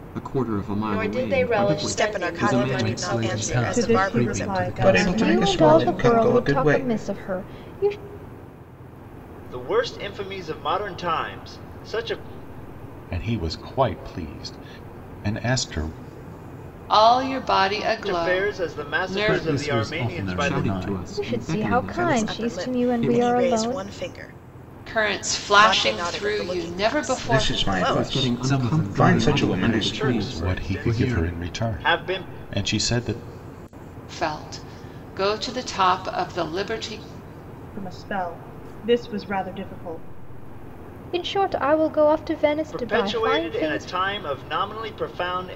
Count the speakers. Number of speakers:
10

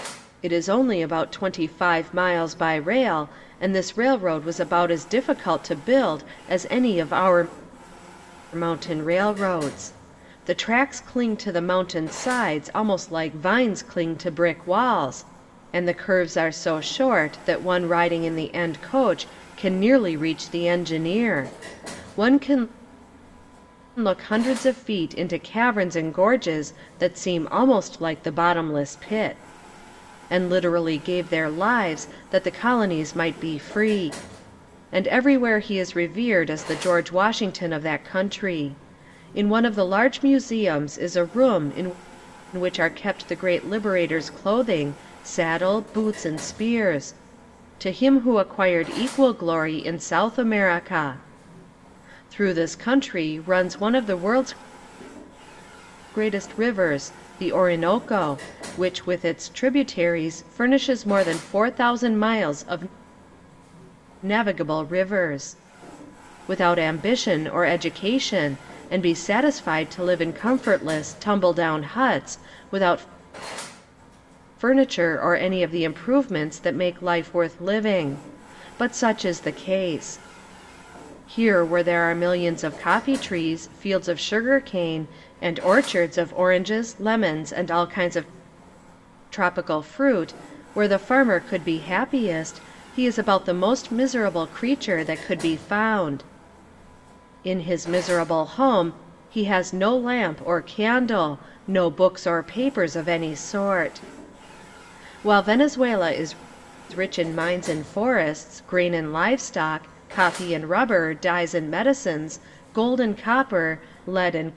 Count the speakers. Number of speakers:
1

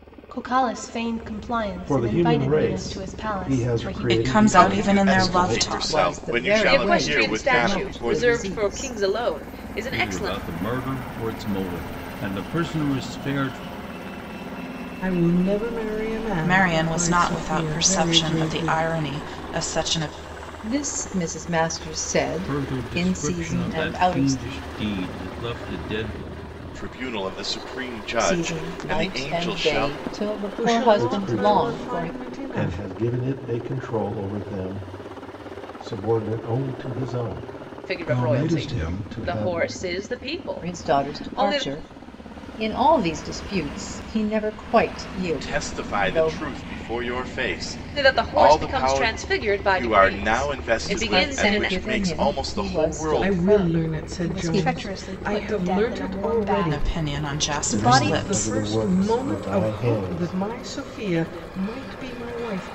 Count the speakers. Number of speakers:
8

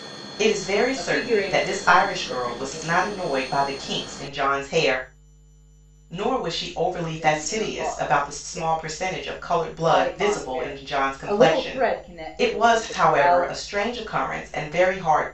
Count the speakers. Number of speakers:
2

